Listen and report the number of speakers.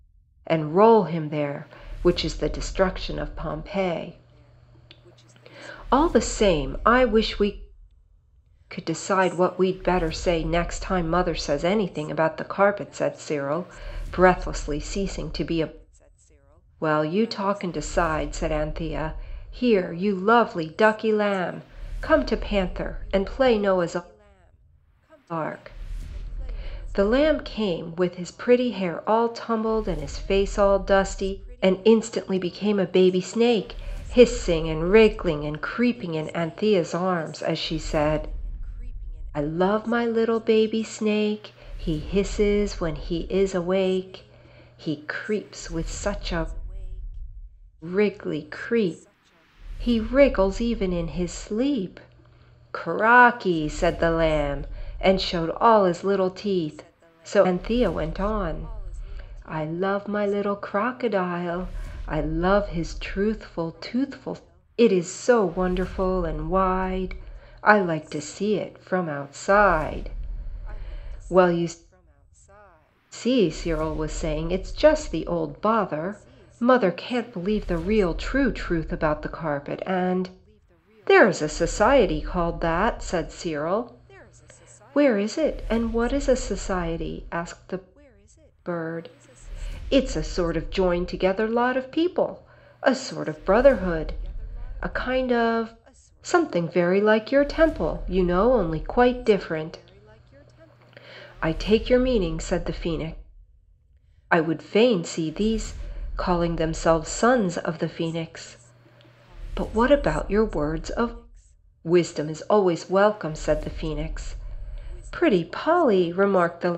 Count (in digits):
1